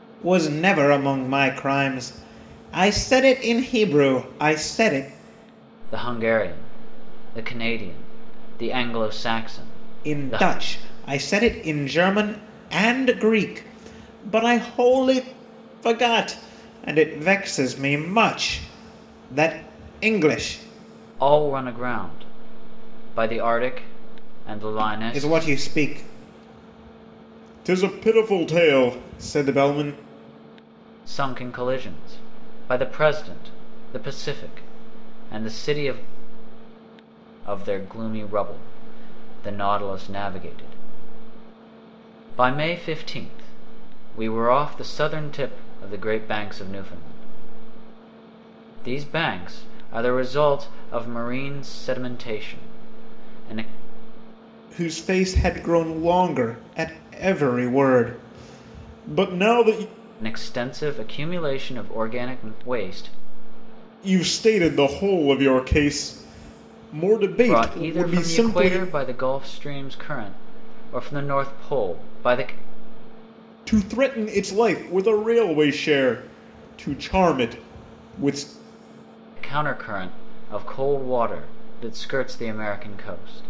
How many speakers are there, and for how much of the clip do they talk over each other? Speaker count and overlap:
2, about 3%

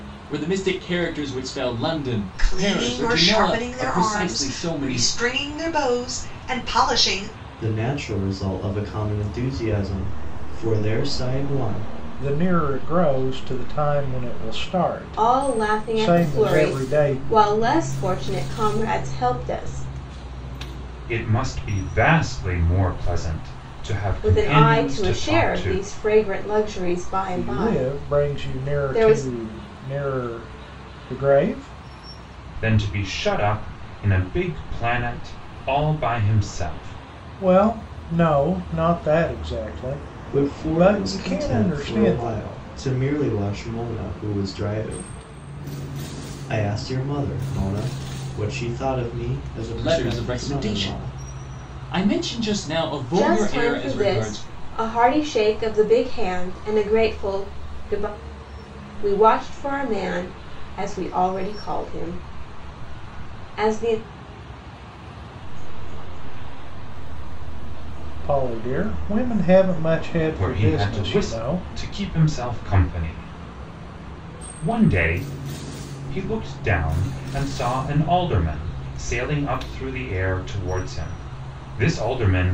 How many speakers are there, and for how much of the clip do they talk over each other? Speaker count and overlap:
7, about 25%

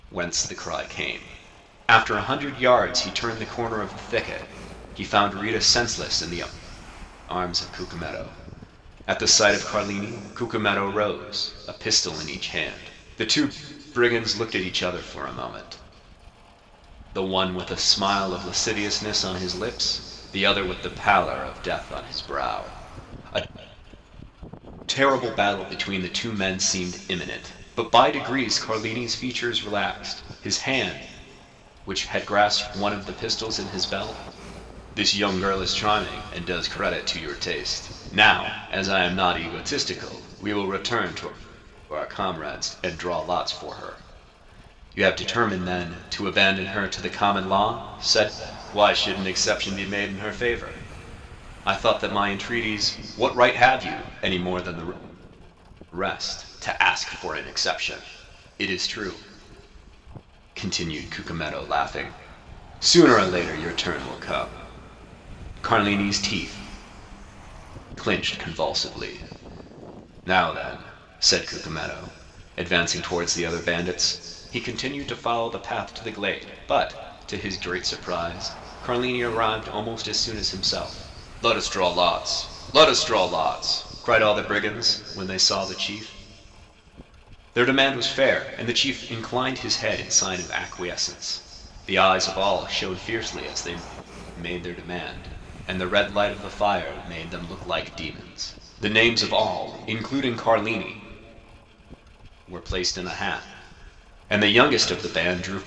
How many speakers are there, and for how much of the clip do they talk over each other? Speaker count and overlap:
1, no overlap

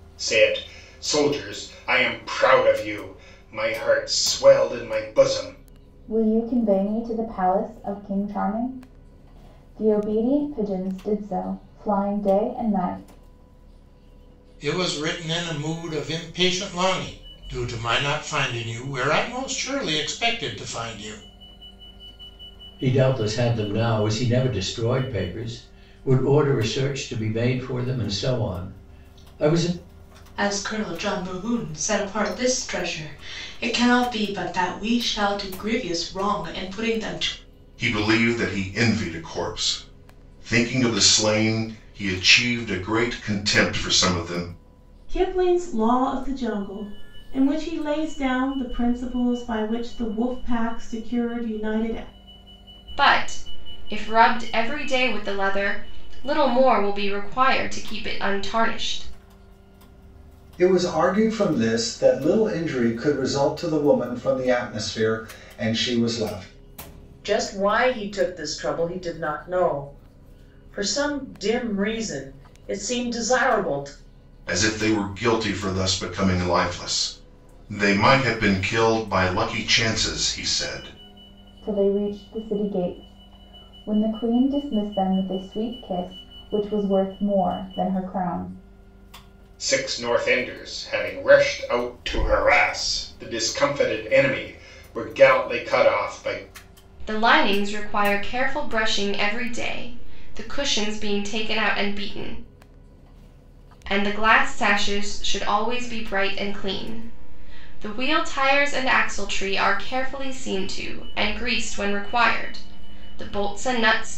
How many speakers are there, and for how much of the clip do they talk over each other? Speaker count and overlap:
10, no overlap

